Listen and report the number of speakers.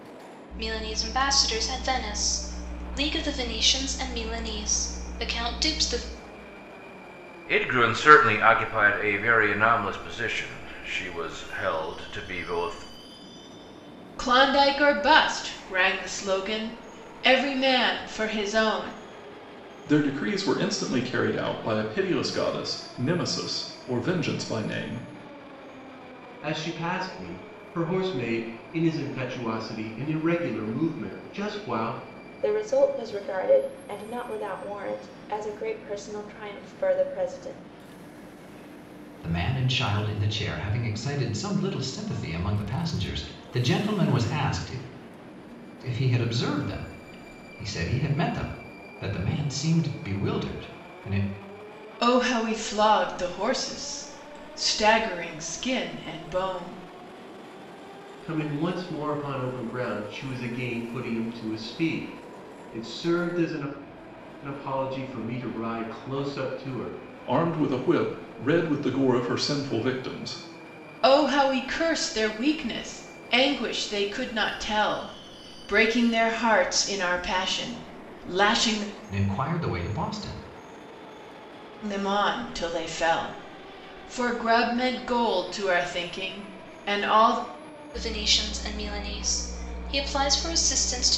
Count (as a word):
seven